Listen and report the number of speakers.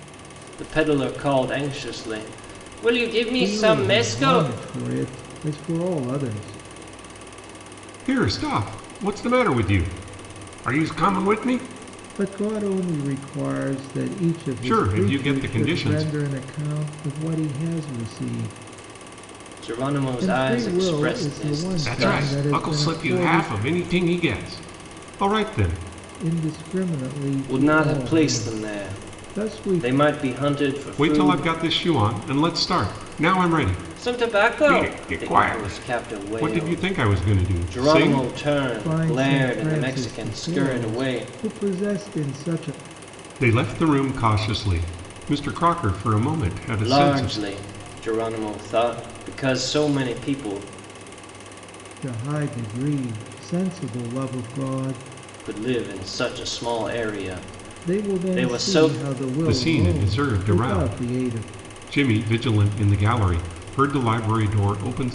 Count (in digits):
3